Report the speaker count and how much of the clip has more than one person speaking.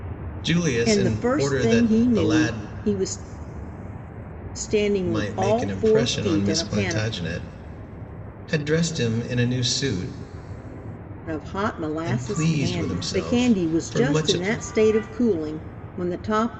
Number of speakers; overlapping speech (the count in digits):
2, about 37%